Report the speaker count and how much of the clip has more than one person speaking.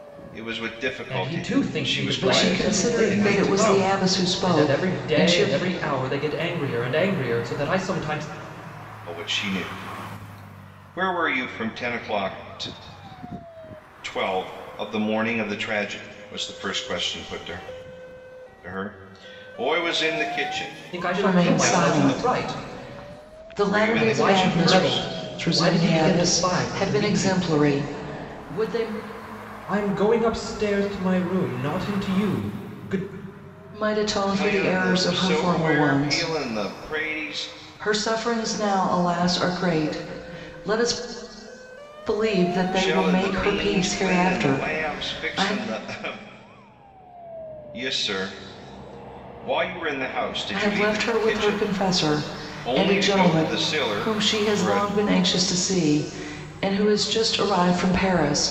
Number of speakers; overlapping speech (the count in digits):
3, about 32%